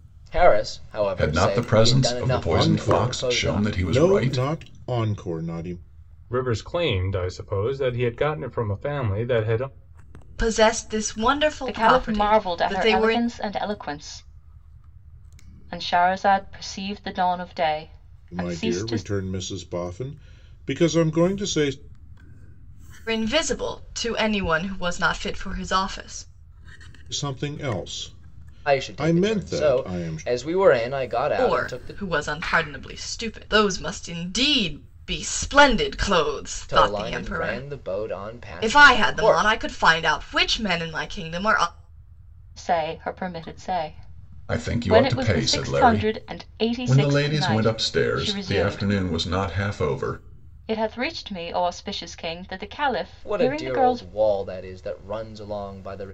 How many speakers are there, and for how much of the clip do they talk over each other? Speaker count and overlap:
6, about 26%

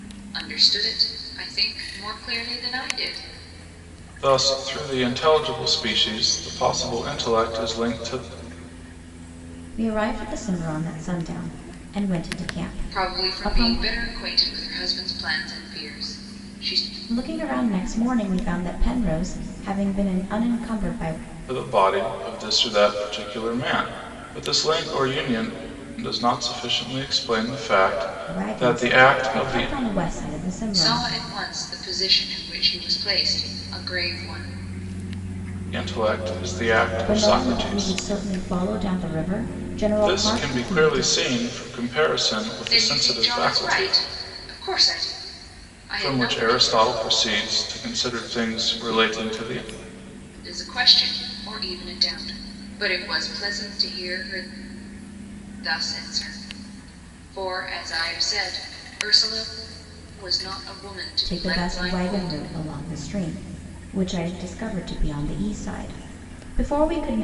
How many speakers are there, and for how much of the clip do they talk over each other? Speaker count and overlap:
3, about 12%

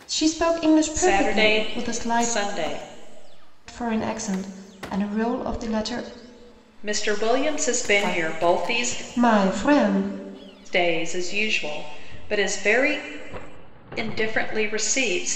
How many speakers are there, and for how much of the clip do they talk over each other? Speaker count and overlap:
2, about 16%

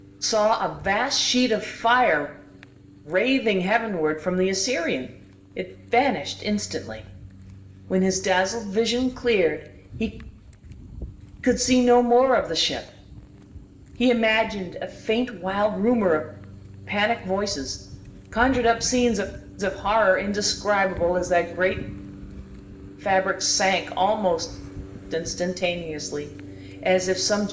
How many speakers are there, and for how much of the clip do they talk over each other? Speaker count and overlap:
1, no overlap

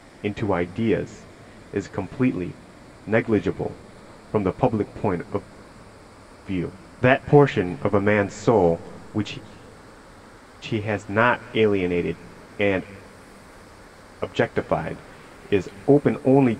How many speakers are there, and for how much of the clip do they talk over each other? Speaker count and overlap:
1, no overlap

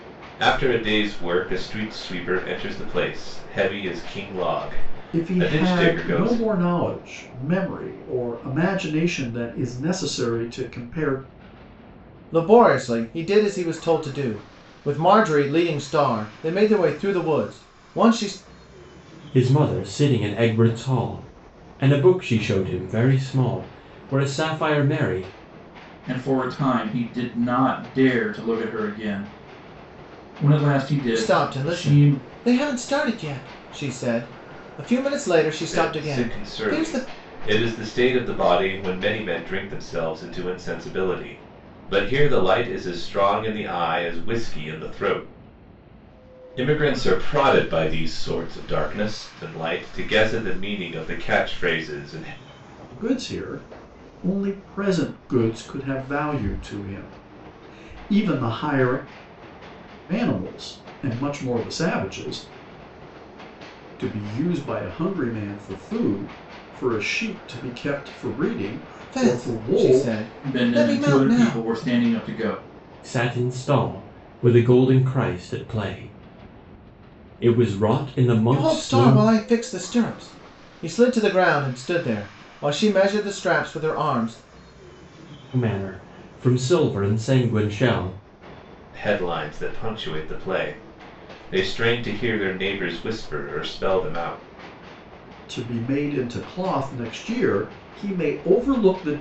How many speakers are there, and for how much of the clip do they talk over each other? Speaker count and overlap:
5, about 7%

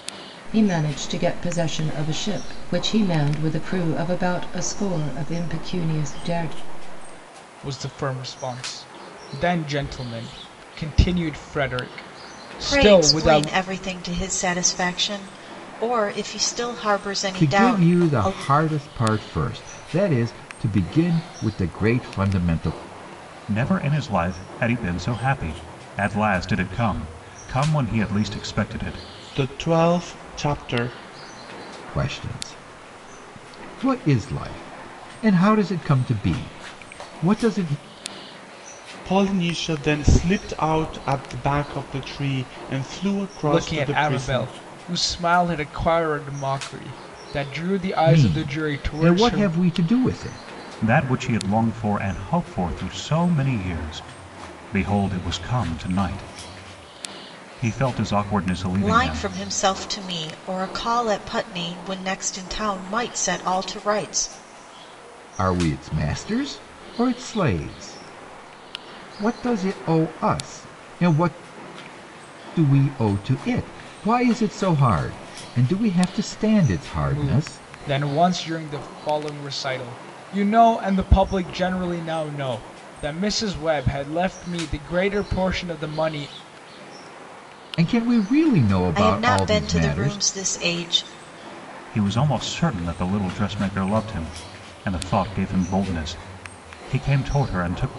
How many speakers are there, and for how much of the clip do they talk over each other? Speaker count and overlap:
6, about 7%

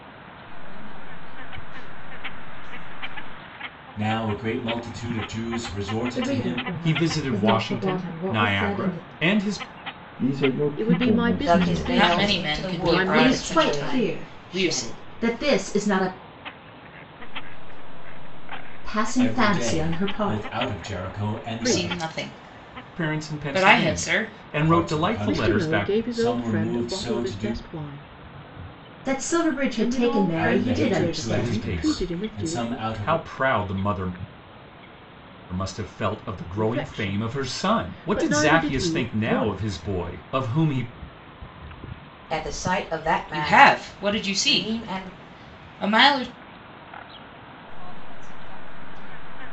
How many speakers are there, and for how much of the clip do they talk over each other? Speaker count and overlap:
9, about 44%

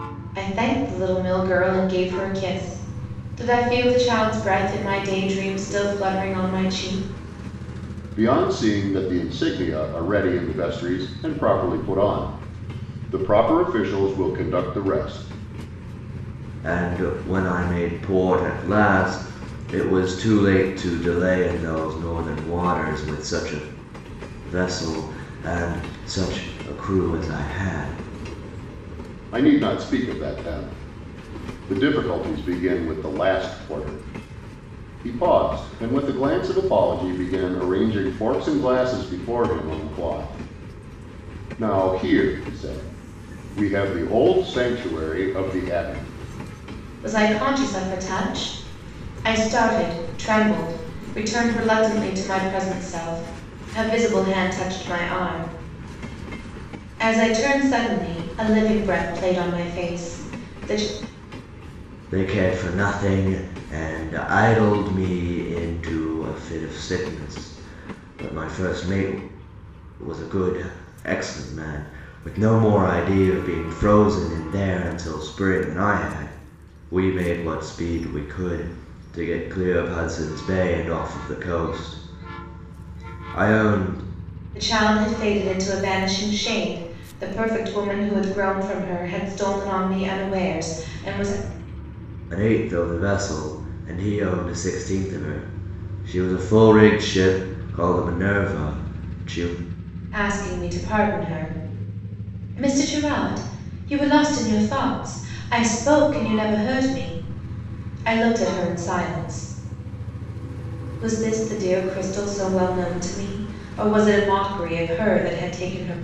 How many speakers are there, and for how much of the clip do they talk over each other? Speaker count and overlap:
3, no overlap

